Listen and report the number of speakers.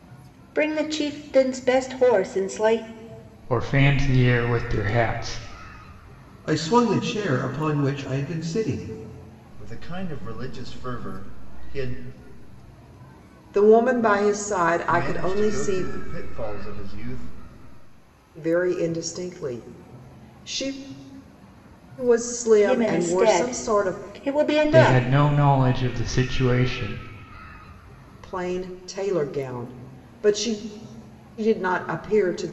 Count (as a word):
five